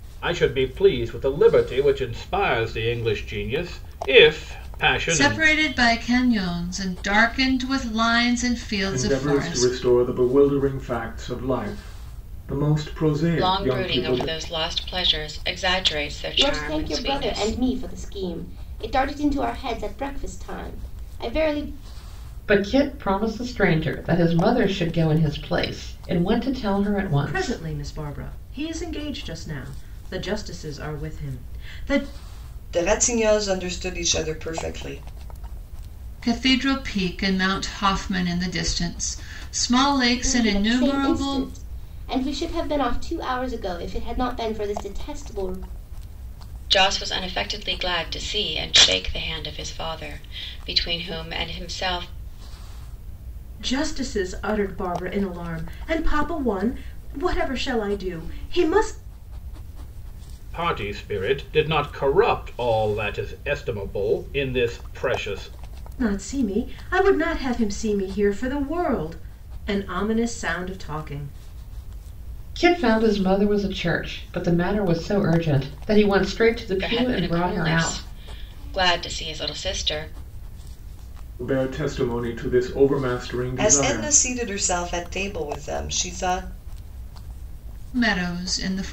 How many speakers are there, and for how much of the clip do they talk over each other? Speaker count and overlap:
8, about 8%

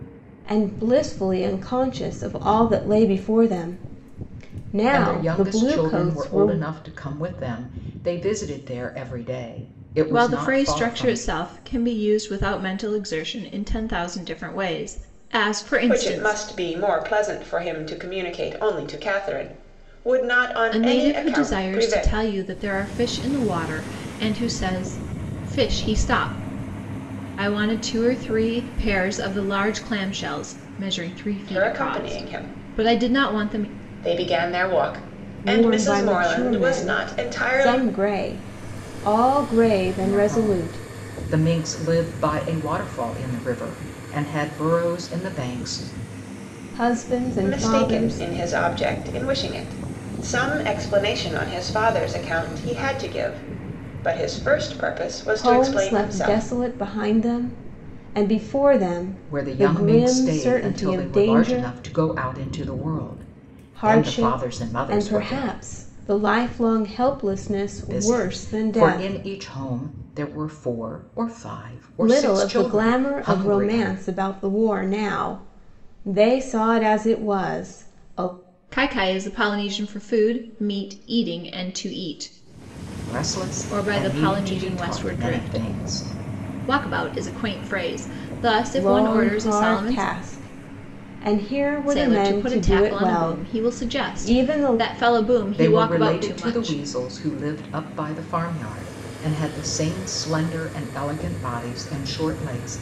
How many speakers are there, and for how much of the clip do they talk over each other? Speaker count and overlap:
4, about 27%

